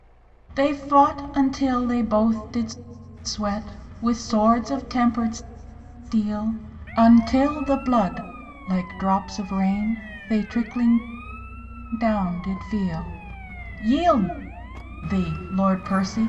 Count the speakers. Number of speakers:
one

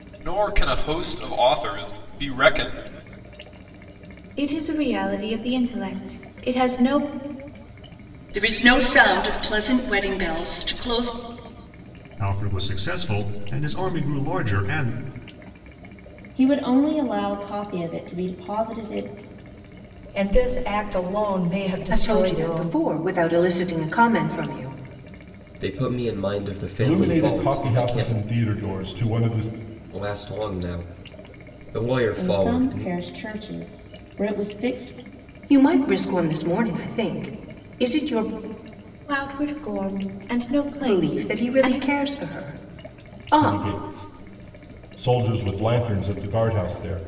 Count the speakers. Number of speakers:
nine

